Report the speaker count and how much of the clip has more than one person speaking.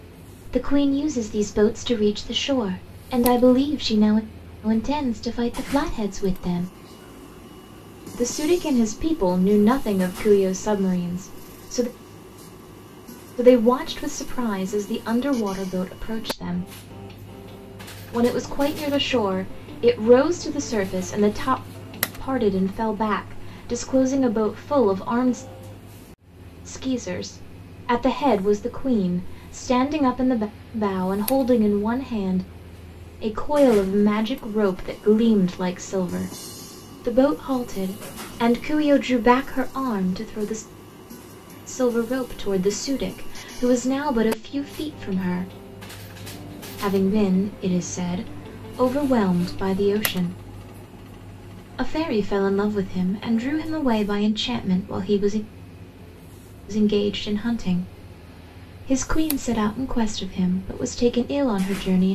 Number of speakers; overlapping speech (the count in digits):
1, no overlap